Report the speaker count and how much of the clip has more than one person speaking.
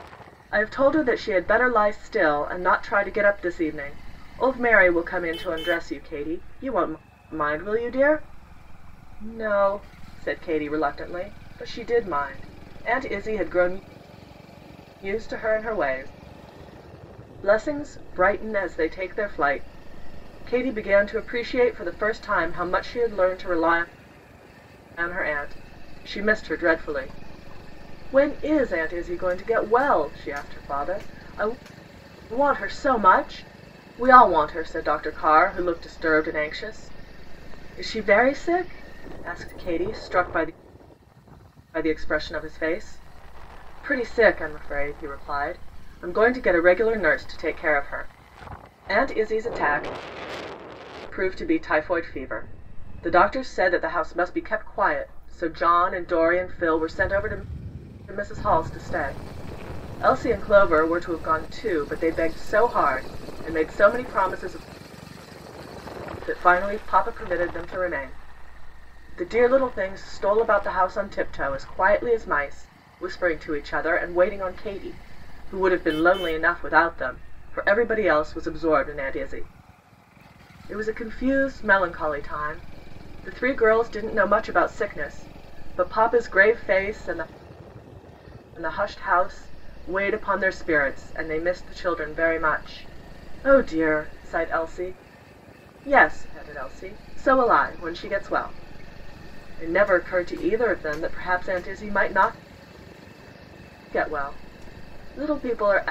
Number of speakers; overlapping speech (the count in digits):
1, no overlap